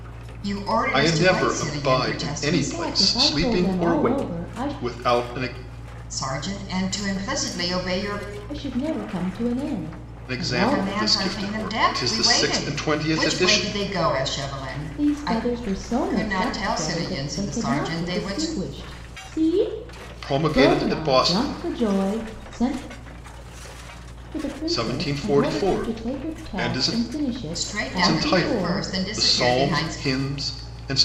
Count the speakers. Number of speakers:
3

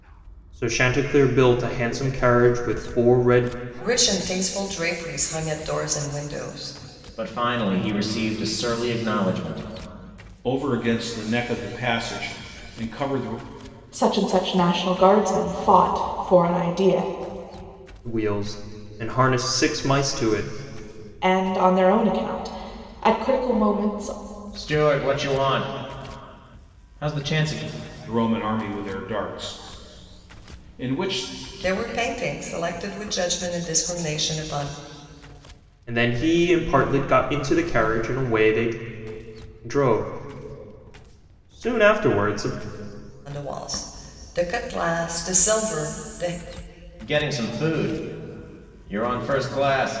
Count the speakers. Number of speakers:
5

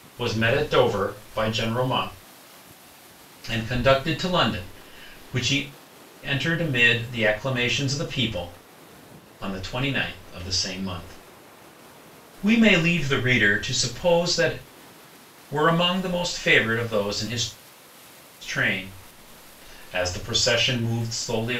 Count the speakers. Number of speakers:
1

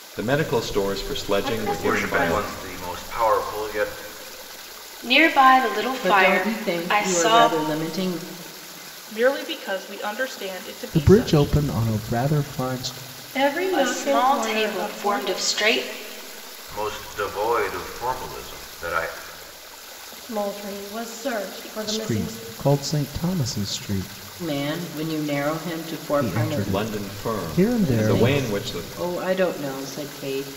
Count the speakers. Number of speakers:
7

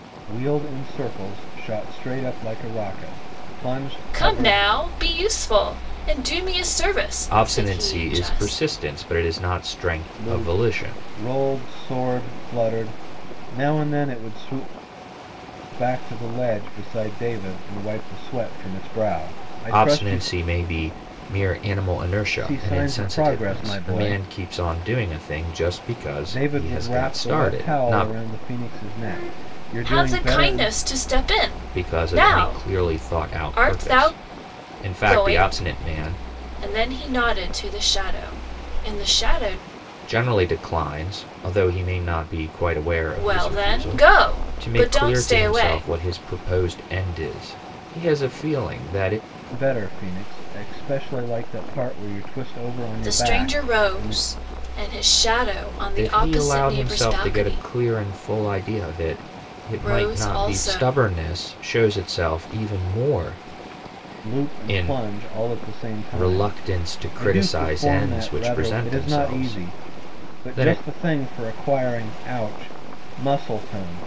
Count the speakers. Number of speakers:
3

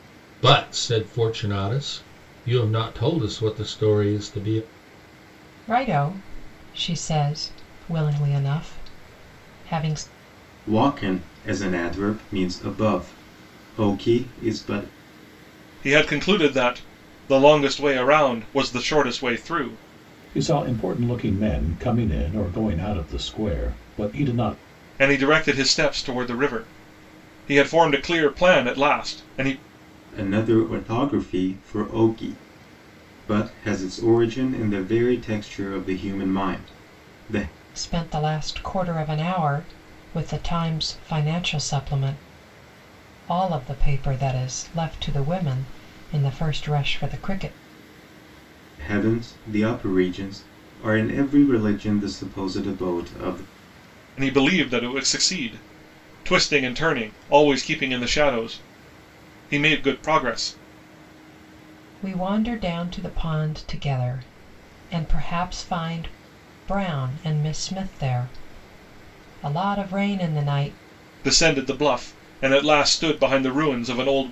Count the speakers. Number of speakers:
5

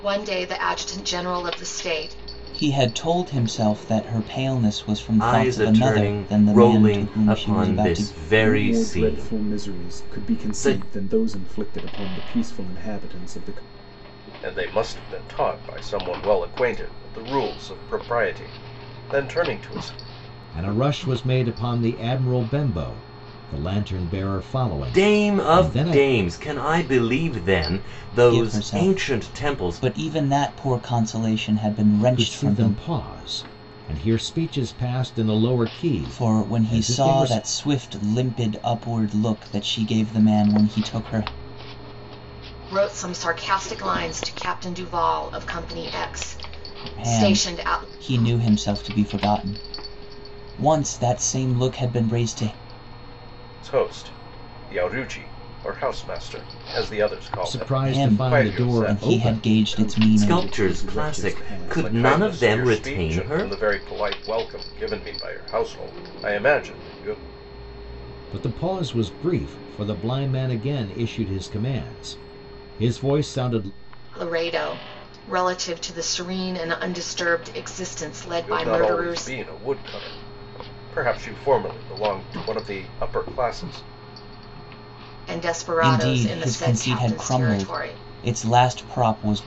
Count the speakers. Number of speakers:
6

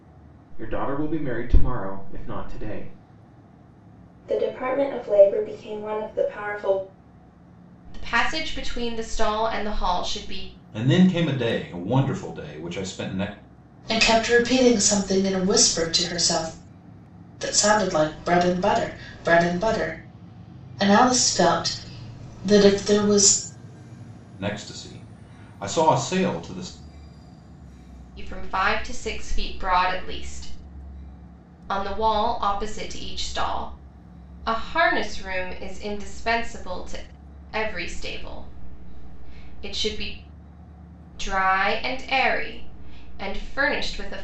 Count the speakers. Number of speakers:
5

